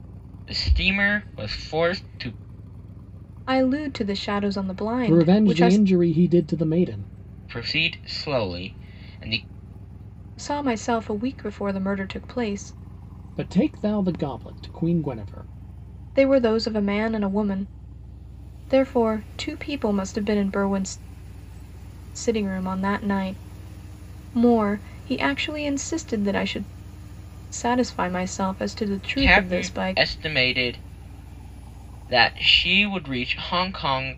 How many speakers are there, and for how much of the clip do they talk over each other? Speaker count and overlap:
3, about 5%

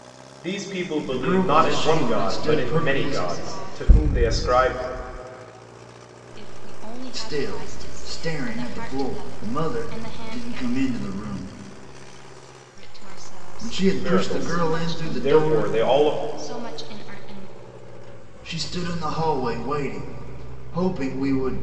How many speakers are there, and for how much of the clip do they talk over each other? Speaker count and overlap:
3, about 42%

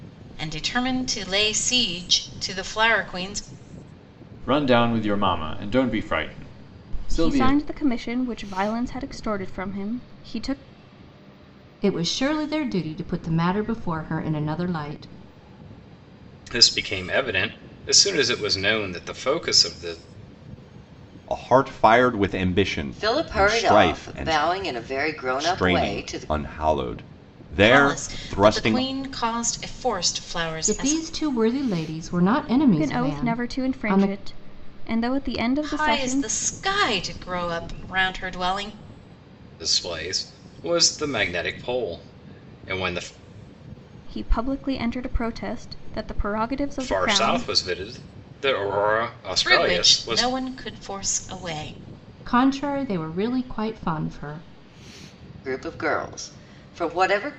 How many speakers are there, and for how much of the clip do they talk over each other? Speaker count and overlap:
7, about 15%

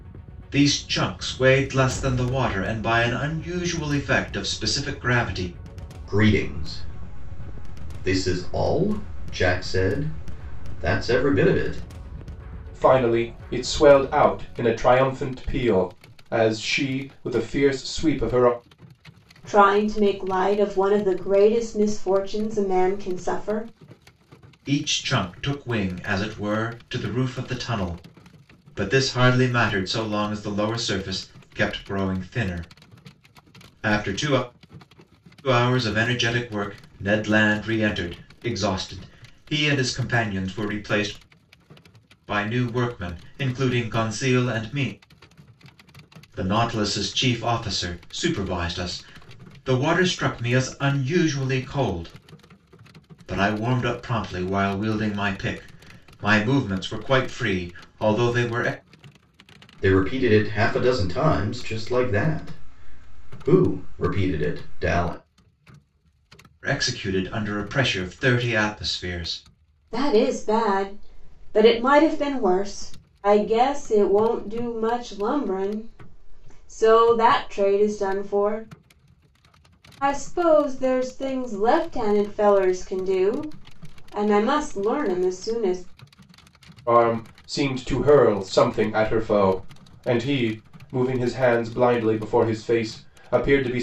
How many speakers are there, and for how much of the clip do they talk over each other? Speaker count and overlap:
4, no overlap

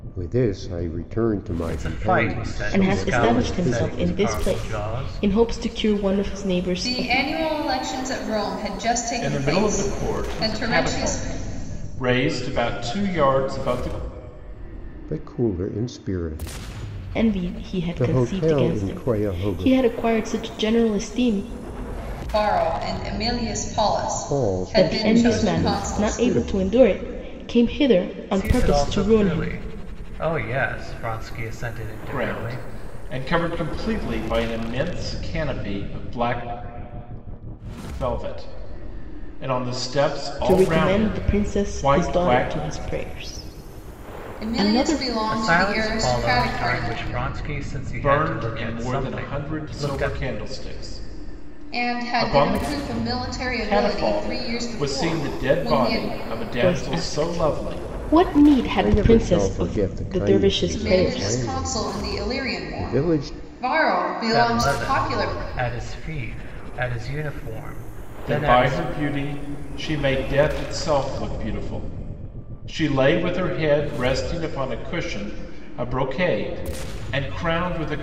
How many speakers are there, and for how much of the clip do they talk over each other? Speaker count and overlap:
5, about 40%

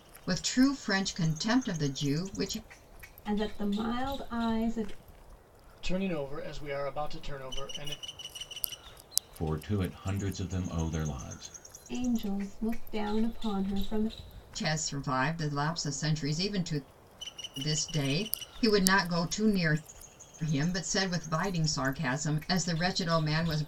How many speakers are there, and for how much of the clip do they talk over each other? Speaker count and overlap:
4, no overlap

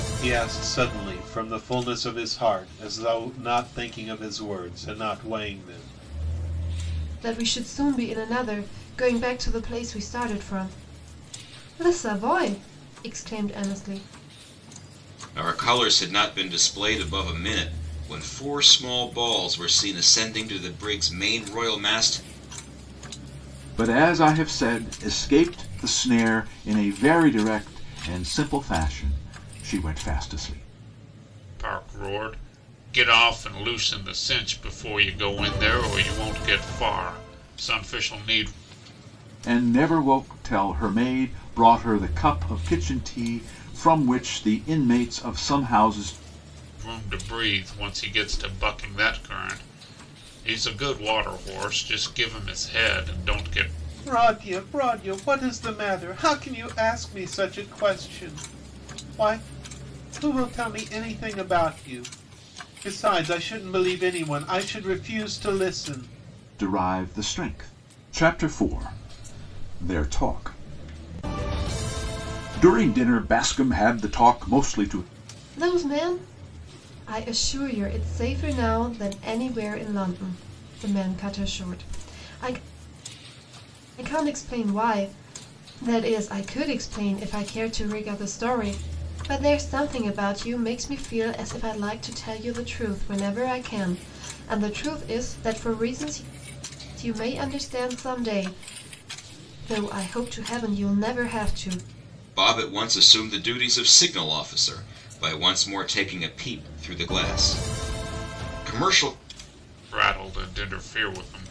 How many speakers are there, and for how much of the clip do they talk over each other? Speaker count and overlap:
5, no overlap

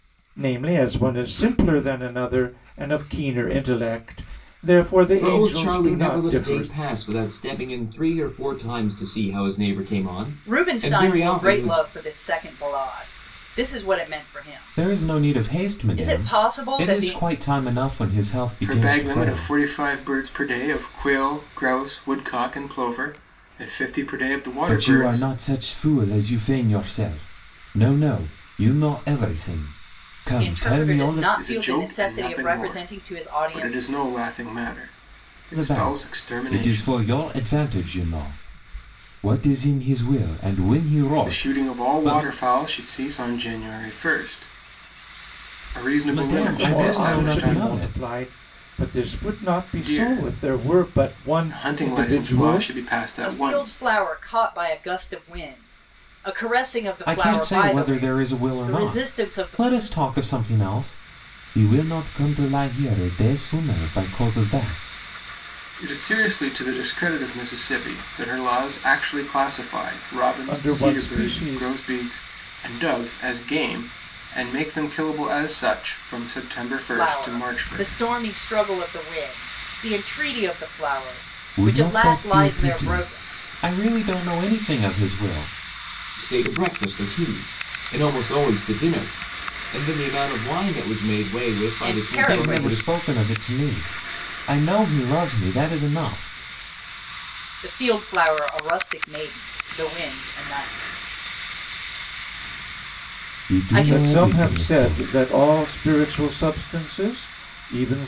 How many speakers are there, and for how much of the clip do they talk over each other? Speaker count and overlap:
5, about 27%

